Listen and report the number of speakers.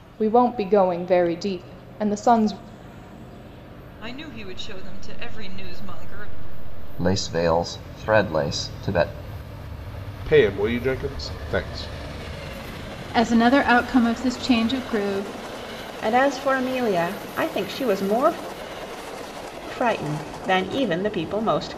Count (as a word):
six